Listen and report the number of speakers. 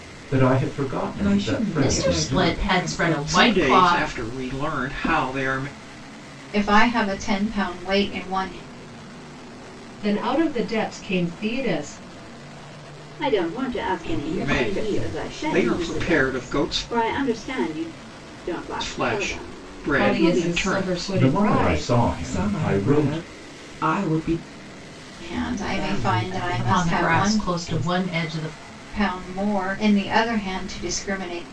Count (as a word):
eight